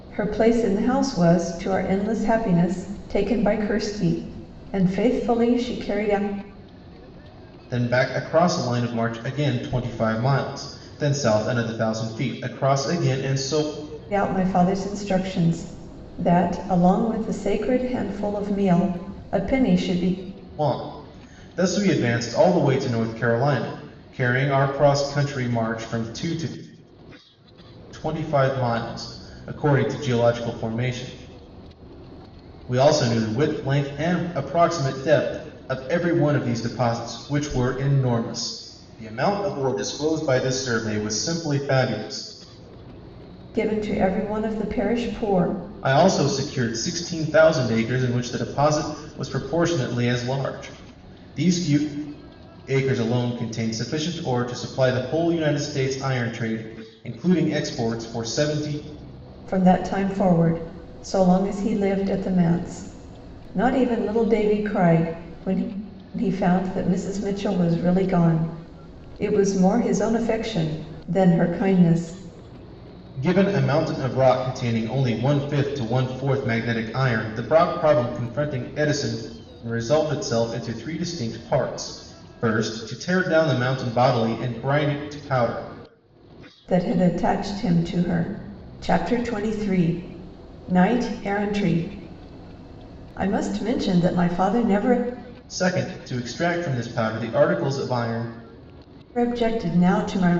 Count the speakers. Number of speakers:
two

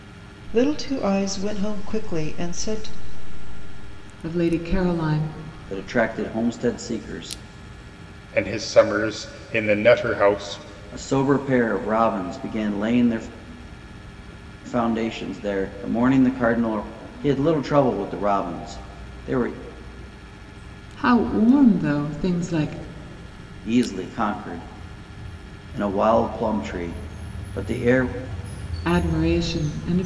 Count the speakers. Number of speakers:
four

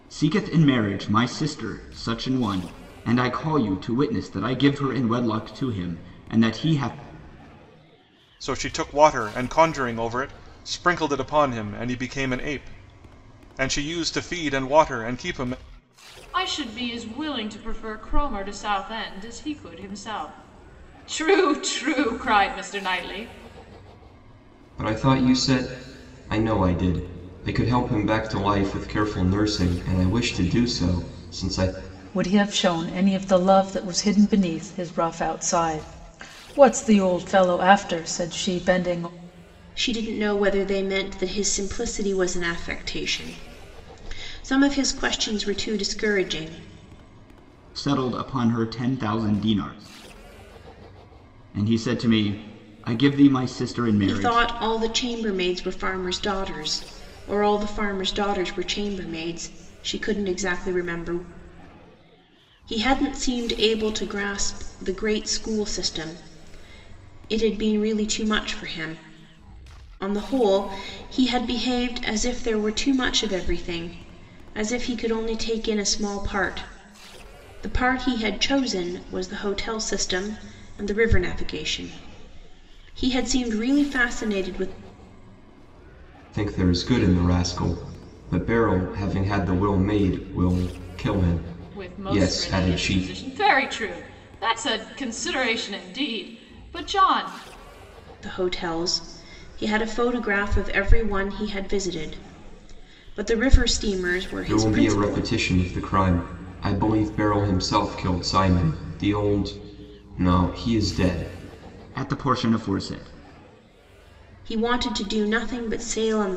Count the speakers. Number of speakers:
six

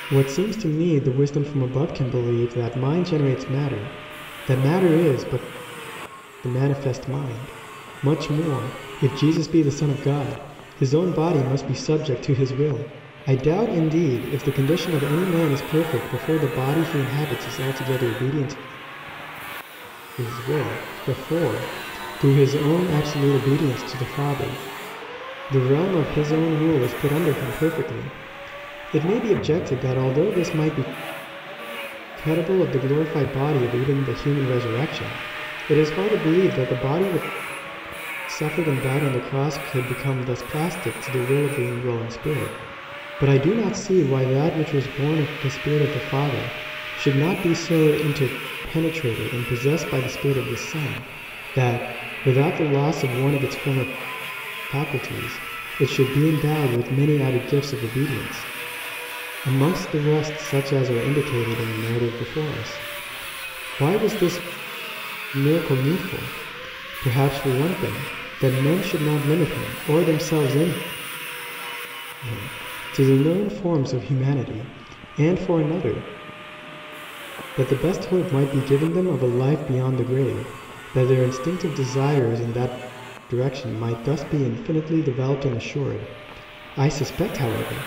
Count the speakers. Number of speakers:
one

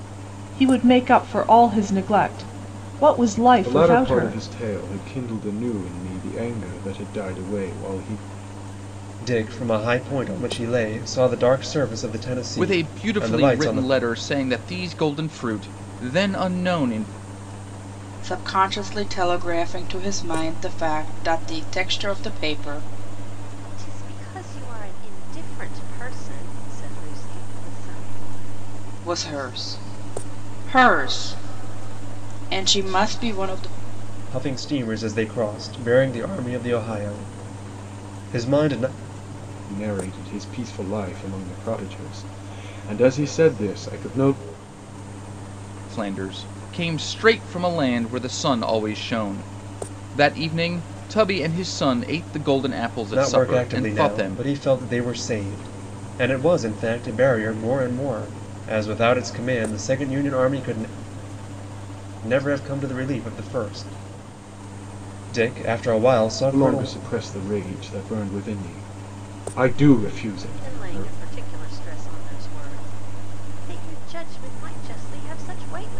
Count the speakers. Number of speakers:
six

